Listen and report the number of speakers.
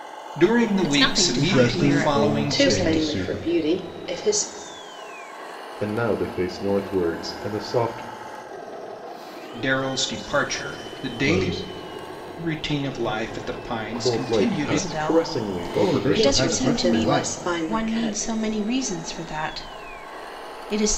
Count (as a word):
five